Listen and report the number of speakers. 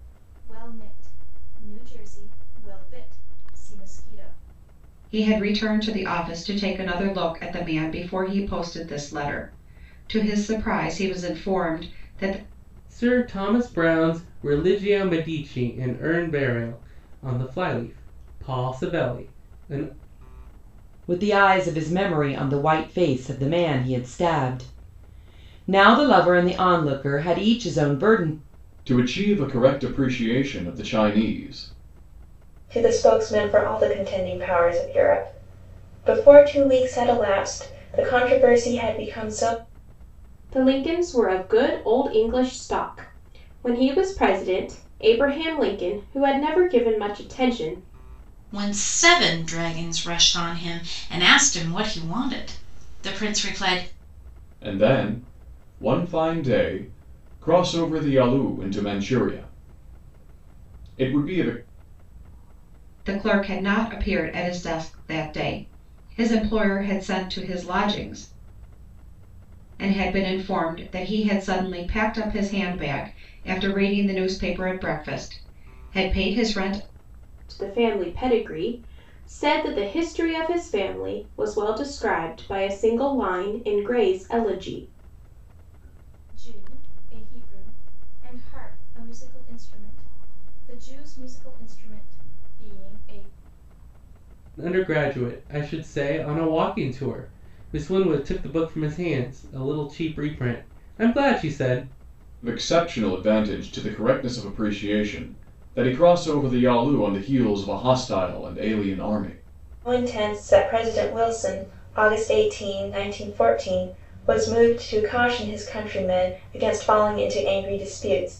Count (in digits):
8